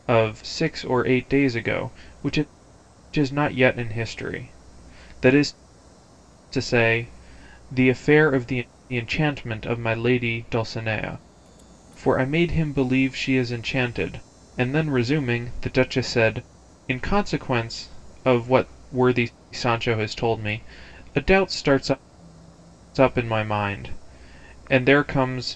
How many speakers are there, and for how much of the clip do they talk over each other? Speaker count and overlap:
1, no overlap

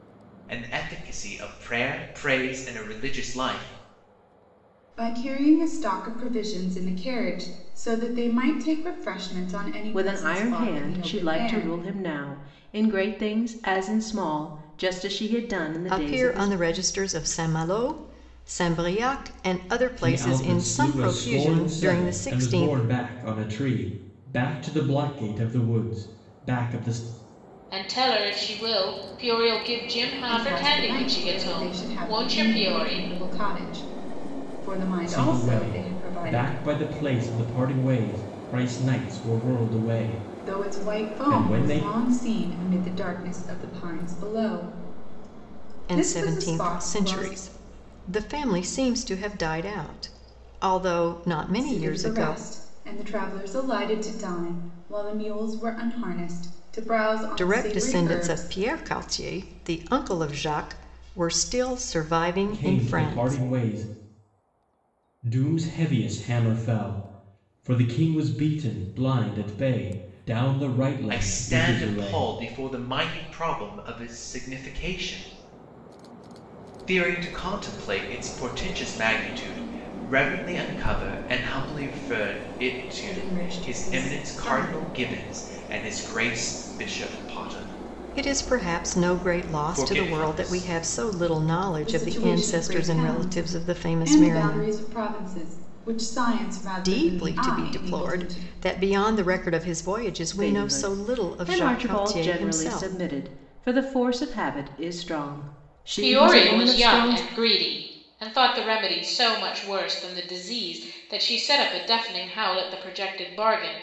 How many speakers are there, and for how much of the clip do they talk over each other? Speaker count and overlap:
6, about 26%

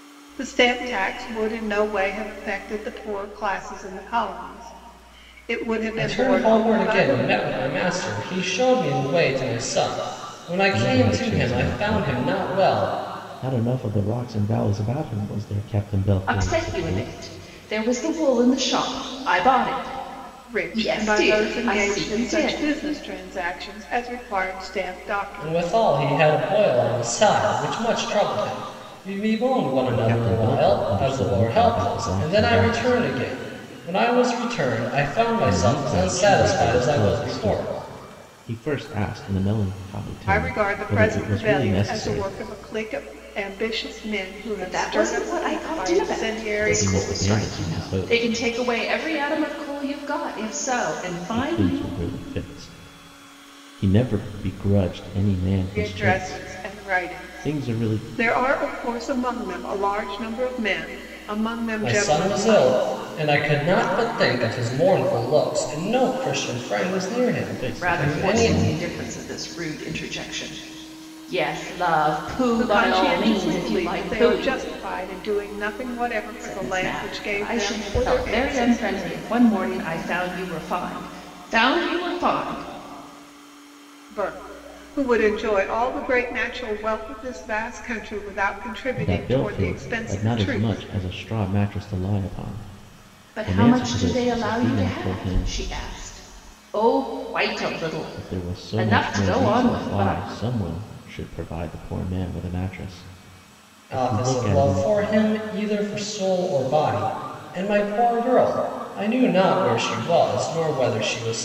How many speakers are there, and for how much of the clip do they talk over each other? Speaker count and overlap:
4, about 32%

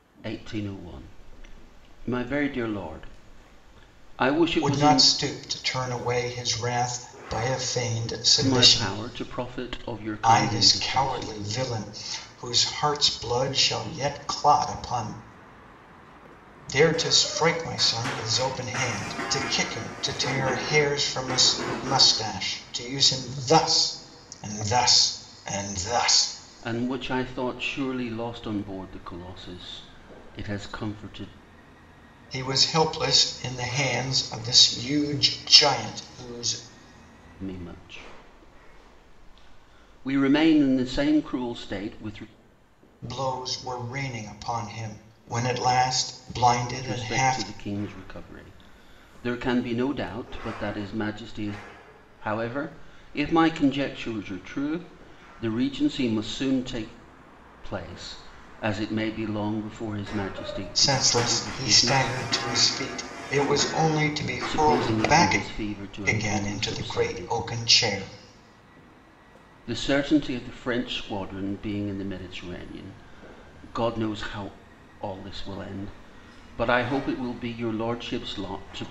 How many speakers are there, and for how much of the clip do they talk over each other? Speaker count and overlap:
2, about 8%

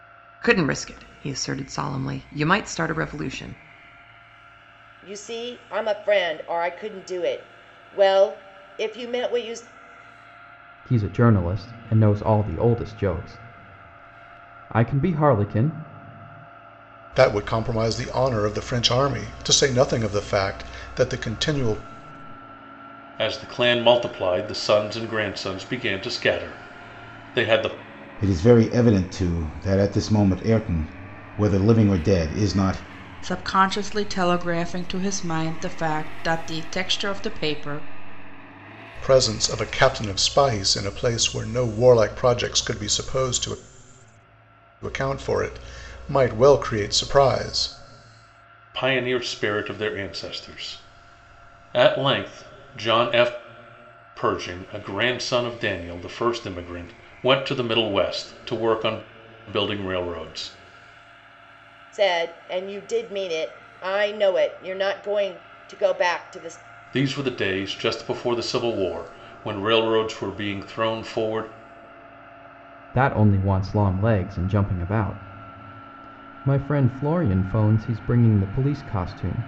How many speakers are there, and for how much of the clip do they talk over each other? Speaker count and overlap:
7, no overlap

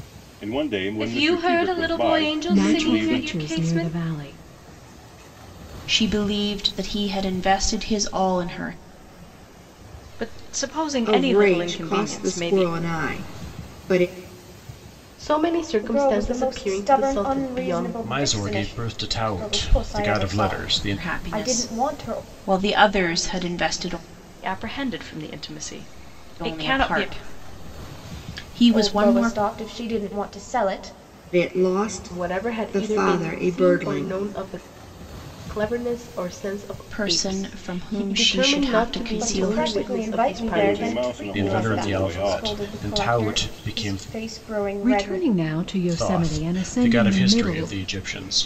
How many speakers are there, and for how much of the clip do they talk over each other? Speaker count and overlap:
9, about 49%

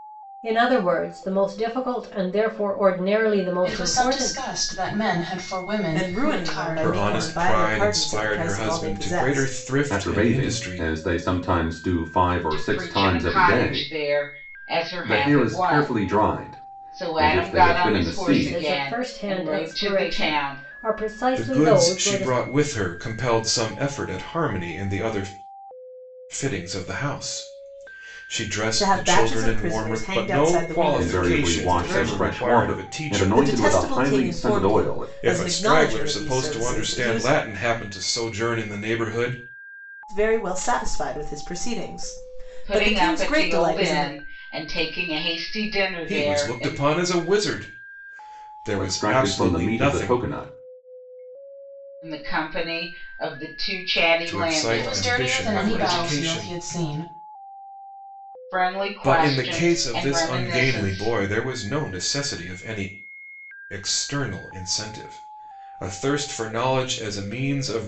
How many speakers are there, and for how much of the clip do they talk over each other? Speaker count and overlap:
6, about 44%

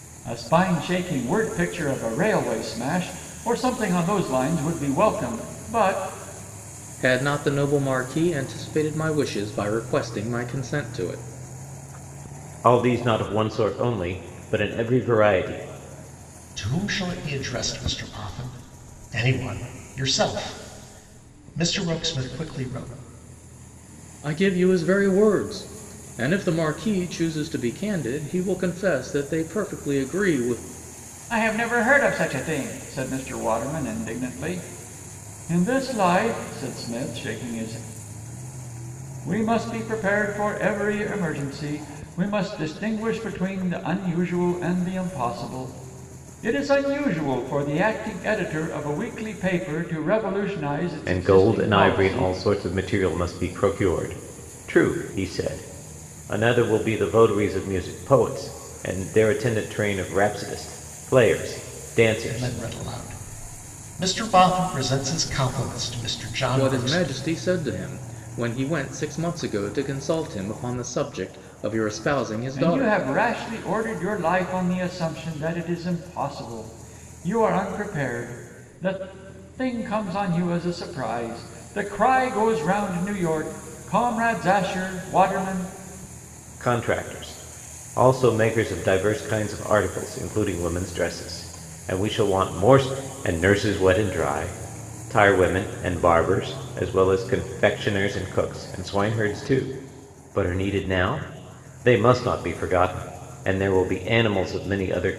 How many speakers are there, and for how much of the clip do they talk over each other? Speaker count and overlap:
4, about 3%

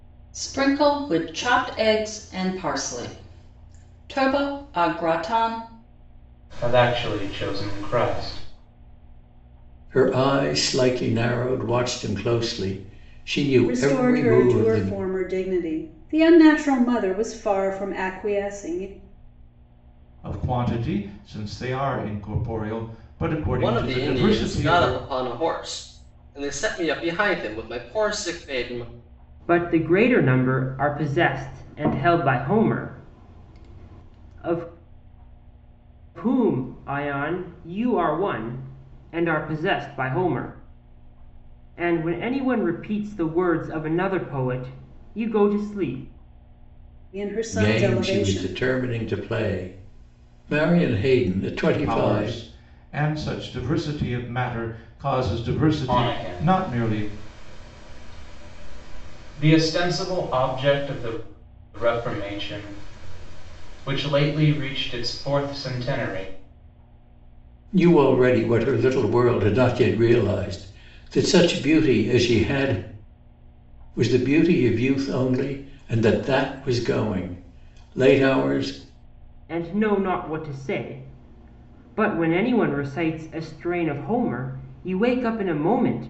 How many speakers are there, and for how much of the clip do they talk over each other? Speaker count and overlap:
7, about 7%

